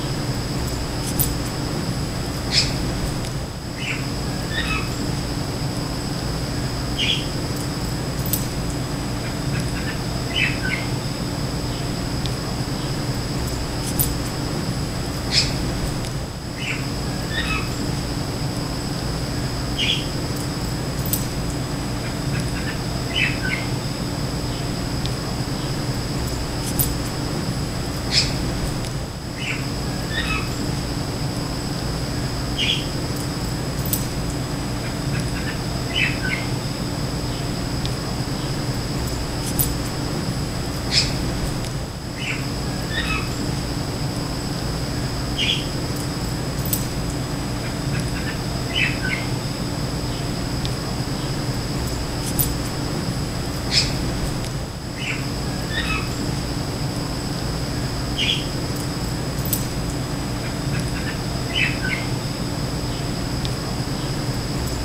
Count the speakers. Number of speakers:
zero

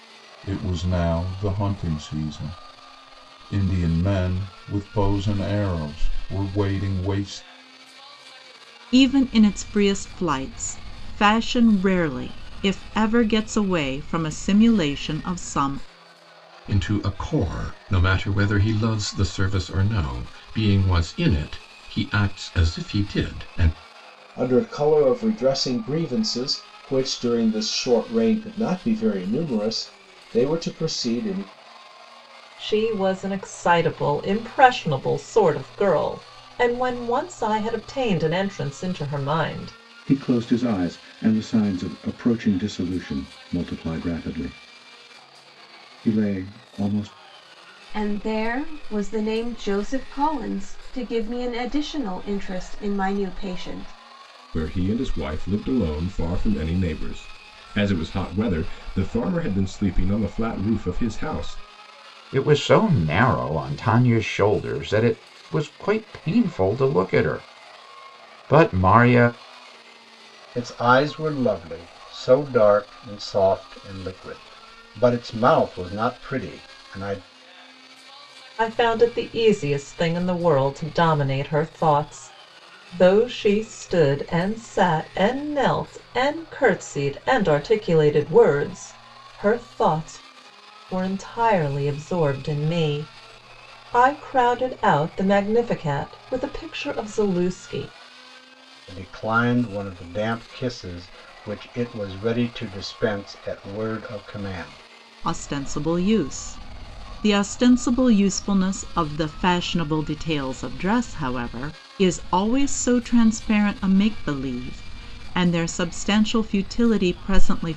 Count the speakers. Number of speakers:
ten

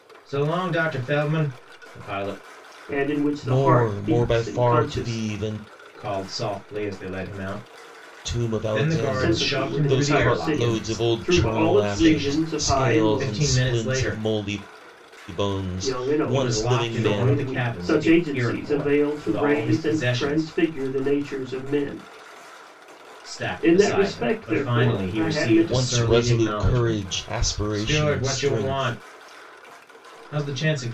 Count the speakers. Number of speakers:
three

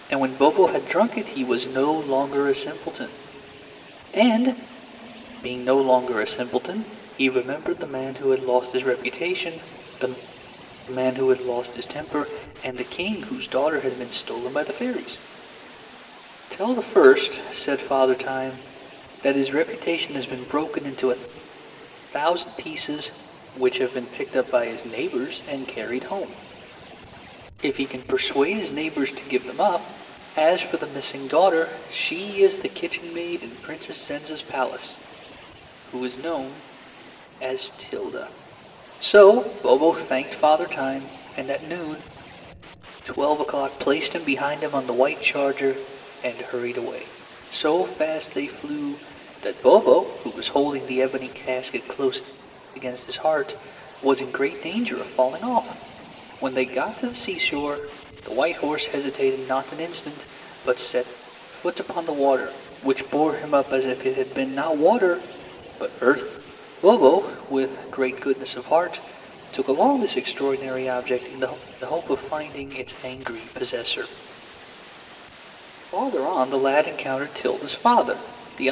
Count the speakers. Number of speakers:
one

